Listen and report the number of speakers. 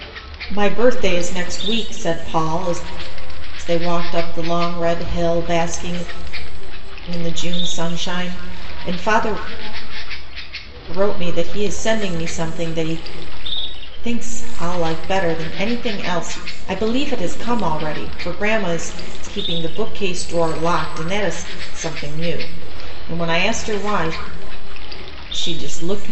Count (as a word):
one